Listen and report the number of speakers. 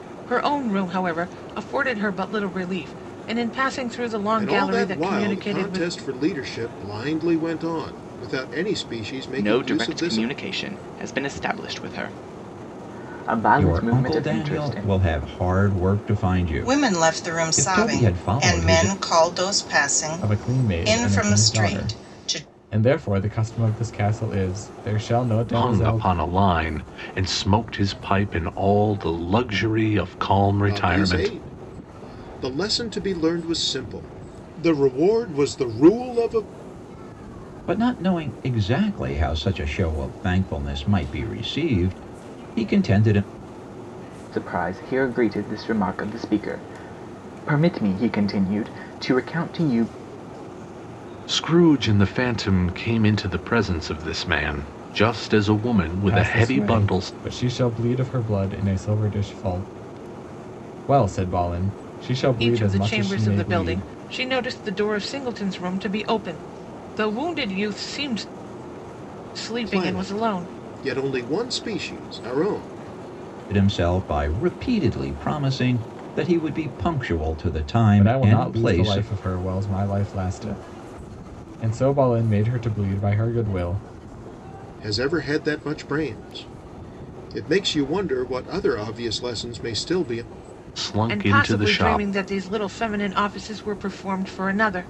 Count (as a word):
seven